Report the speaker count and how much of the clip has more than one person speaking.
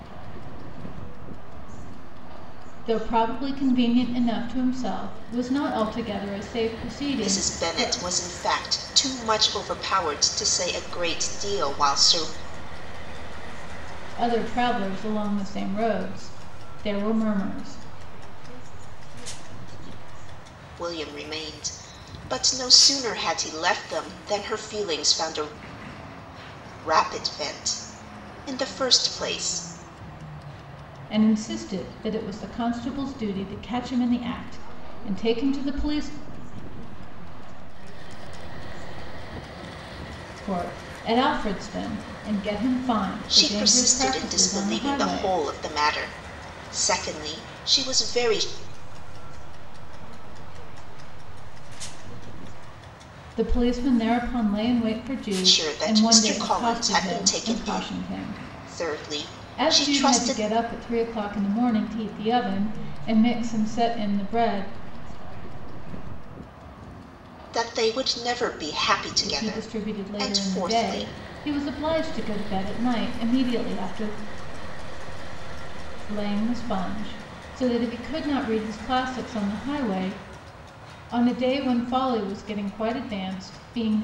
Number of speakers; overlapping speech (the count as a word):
three, about 29%